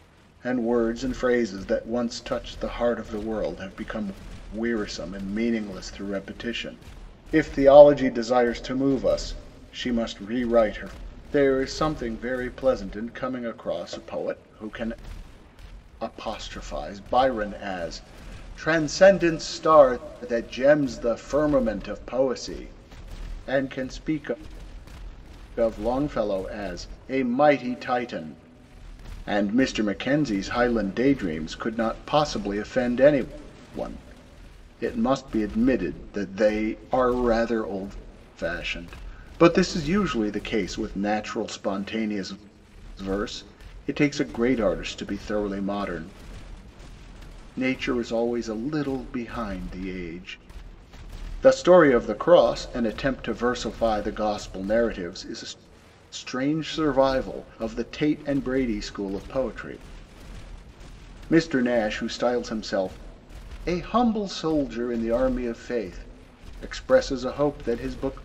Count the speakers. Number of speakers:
1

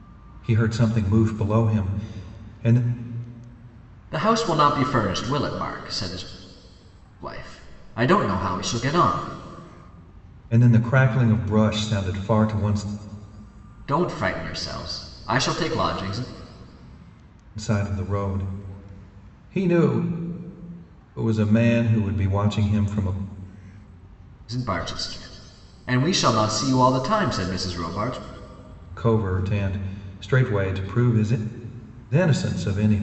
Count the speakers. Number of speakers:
2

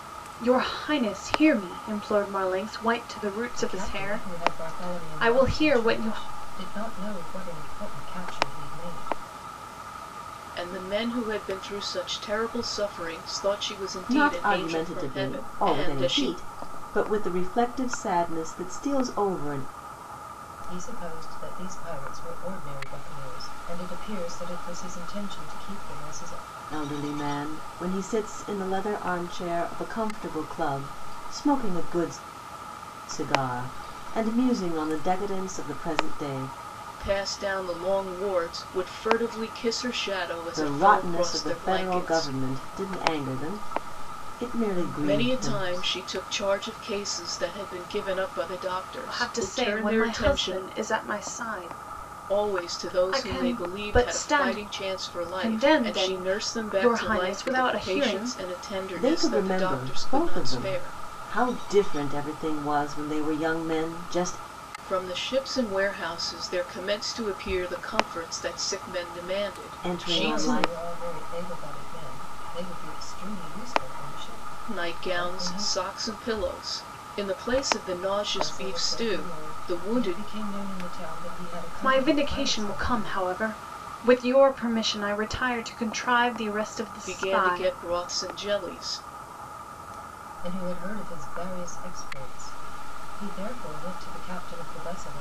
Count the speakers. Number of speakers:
4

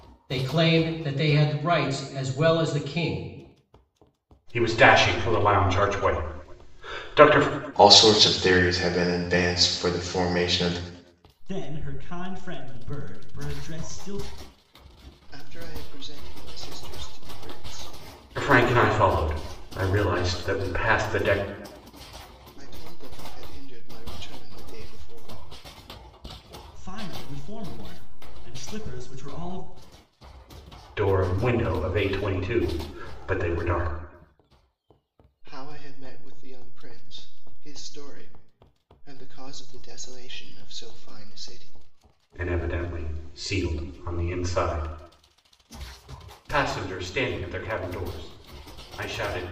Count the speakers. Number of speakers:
5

